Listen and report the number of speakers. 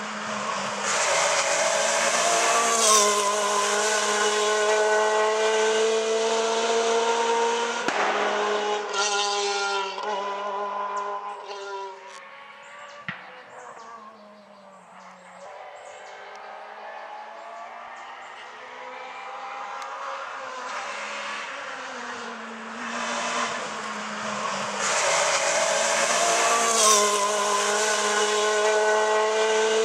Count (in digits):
0